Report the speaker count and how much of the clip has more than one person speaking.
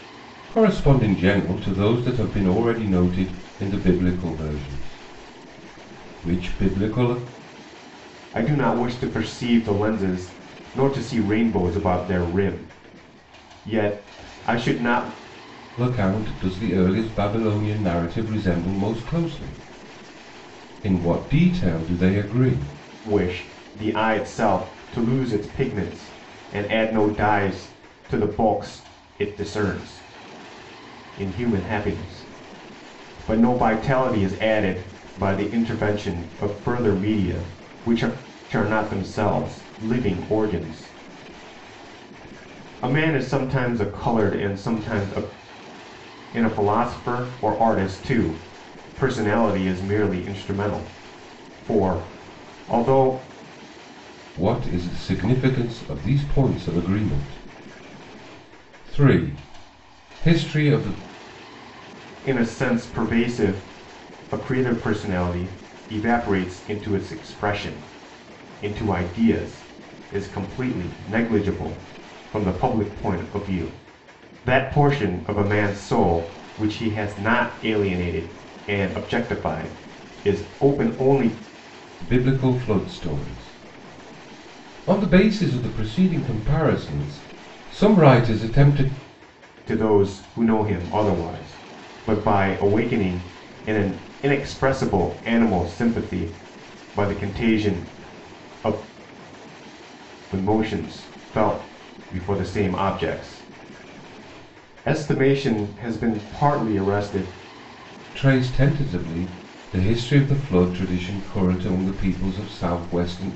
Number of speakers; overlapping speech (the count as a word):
two, no overlap